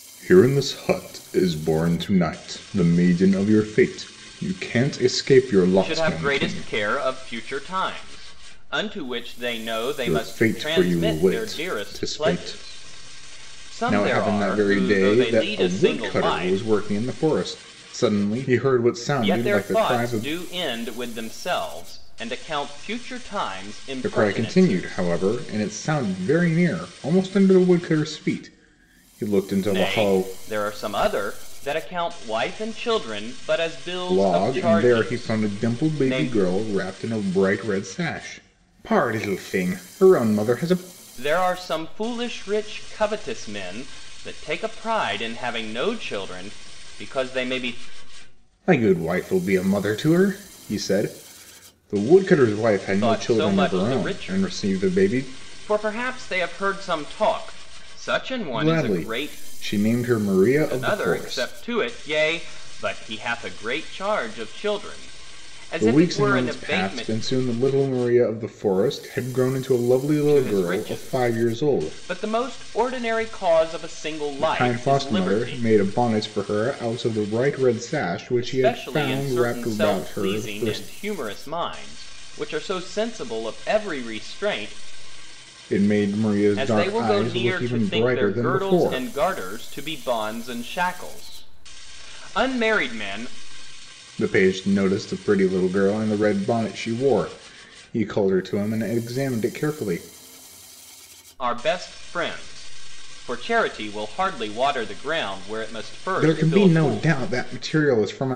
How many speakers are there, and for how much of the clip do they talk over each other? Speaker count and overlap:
two, about 24%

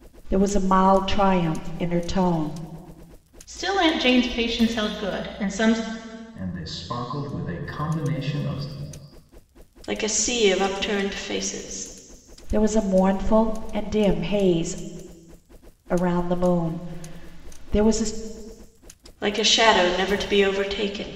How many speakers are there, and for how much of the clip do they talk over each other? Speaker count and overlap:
four, no overlap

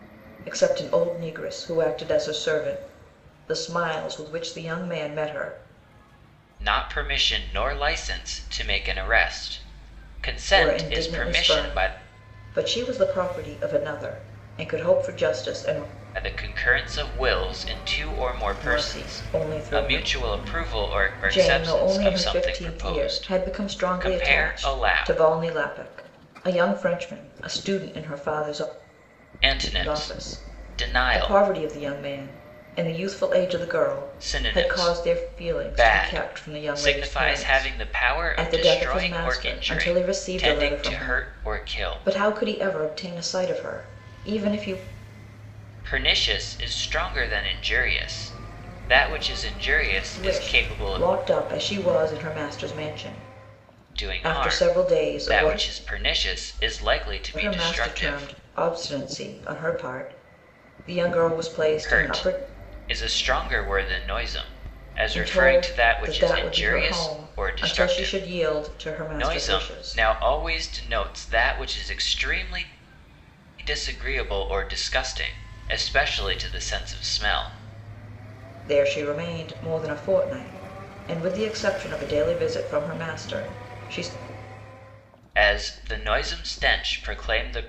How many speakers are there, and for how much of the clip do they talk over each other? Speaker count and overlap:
two, about 29%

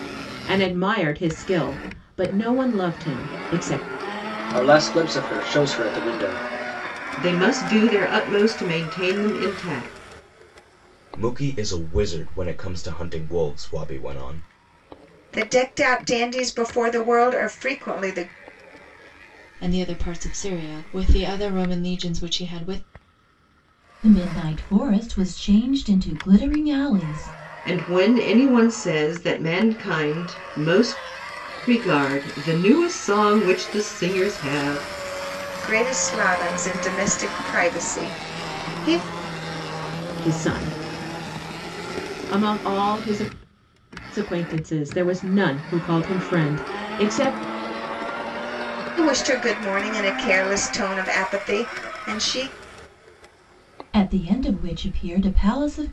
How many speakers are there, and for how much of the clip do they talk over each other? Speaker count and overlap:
seven, no overlap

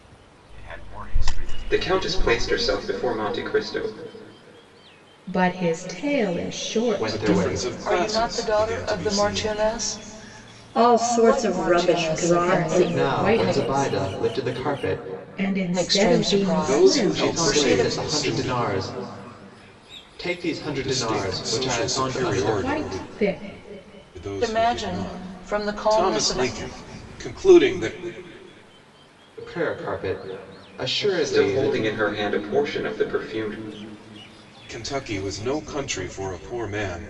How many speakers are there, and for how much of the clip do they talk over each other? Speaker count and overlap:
seven, about 37%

